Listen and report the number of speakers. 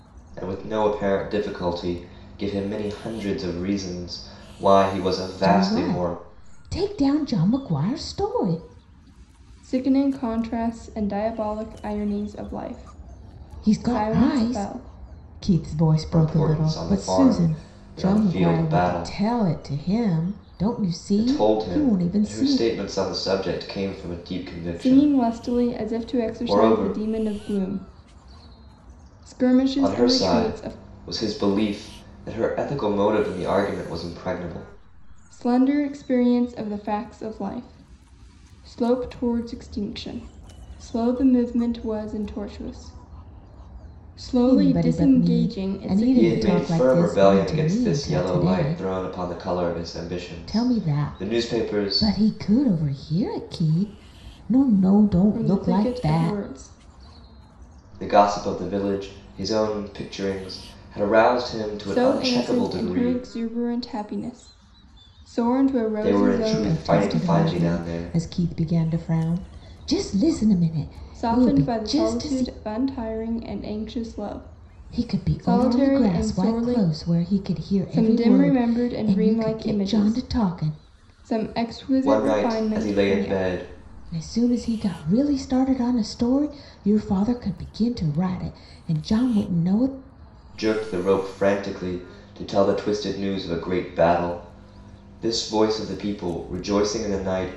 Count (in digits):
3